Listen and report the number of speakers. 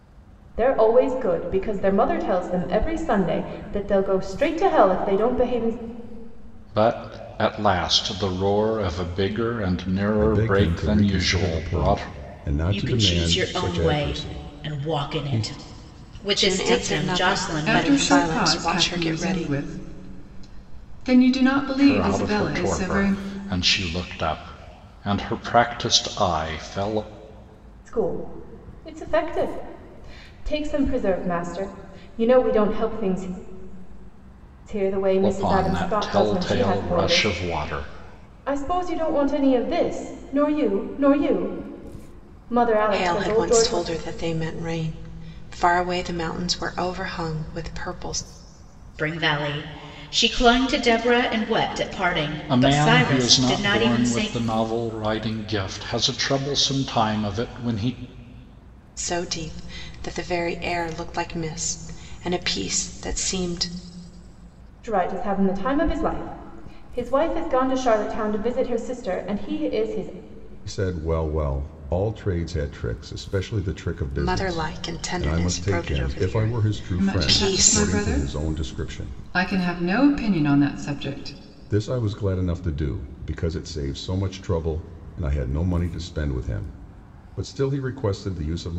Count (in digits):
6